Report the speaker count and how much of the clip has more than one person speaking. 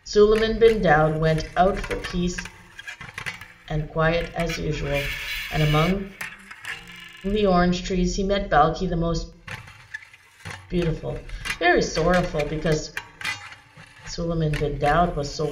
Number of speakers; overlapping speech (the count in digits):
1, no overlap